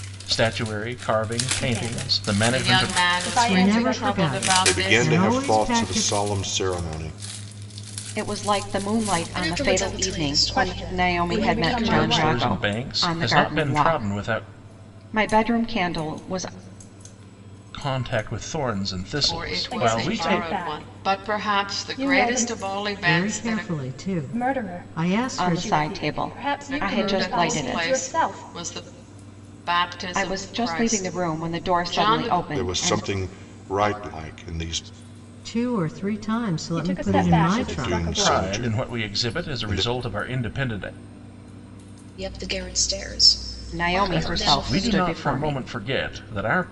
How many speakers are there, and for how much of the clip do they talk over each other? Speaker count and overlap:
seven, about 55%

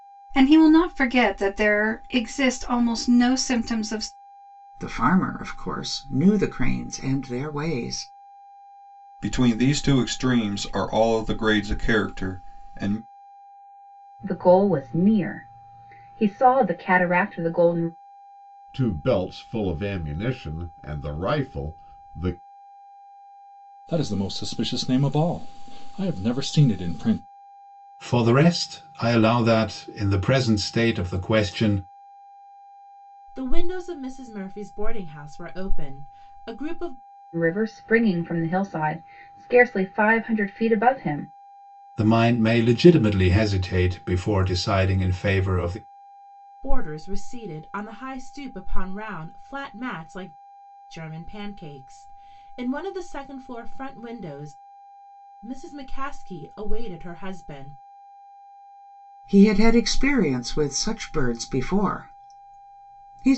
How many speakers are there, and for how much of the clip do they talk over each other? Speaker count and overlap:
eight, no overlap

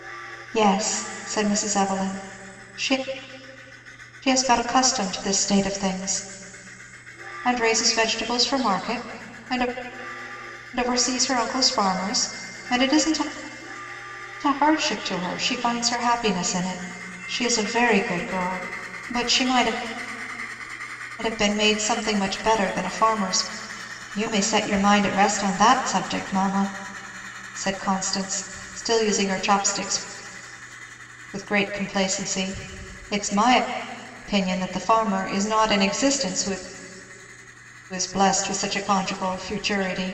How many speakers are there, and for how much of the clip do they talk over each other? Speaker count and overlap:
one, no overlap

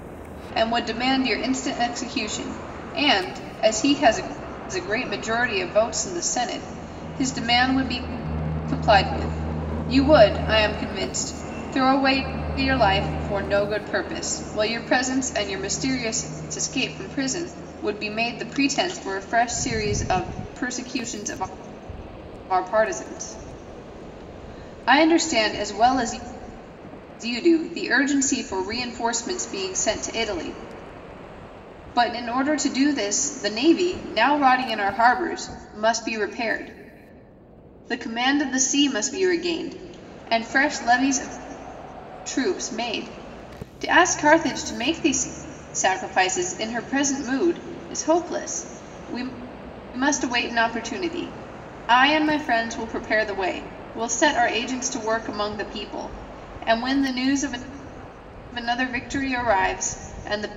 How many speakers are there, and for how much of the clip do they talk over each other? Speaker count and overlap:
one, no overlap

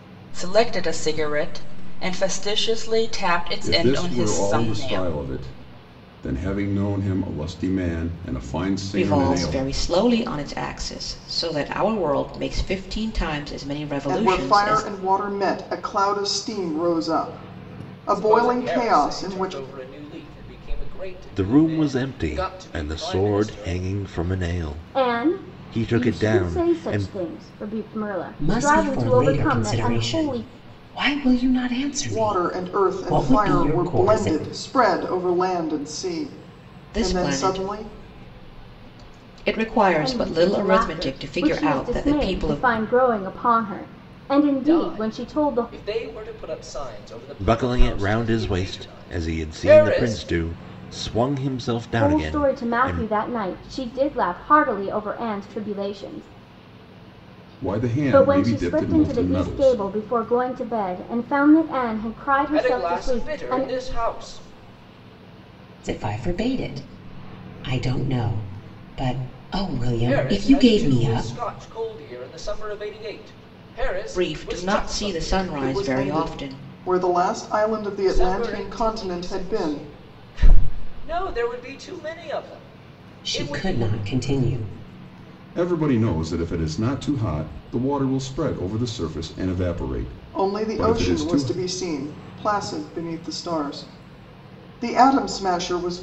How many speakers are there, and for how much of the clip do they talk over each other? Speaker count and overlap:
eight, about 35%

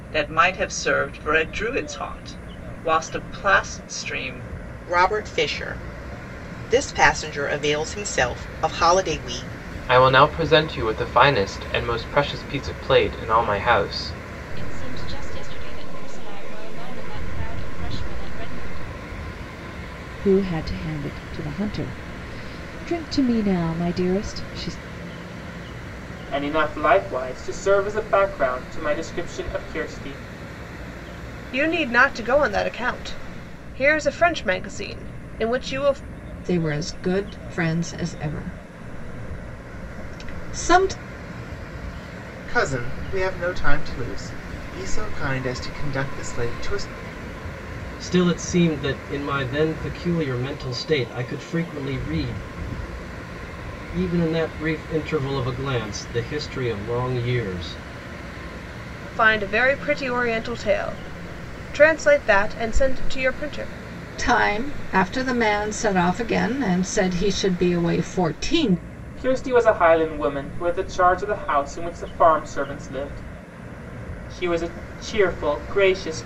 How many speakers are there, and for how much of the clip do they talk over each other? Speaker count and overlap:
ten, no overlap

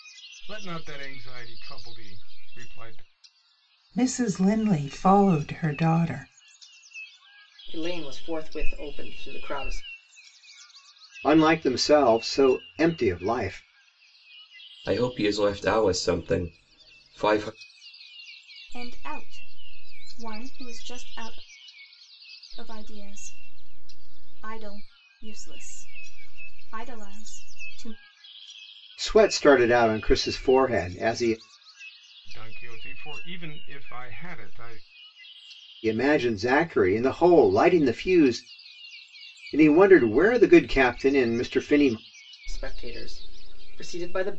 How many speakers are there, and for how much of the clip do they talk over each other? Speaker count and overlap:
six, no overlap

